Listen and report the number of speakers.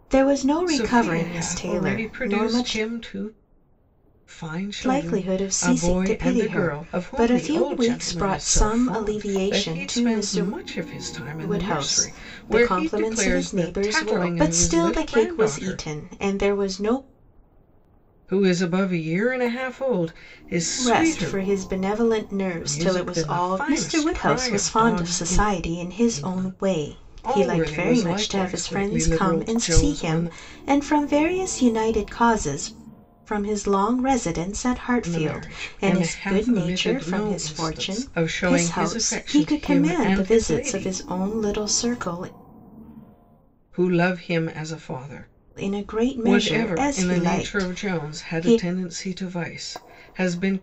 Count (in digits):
2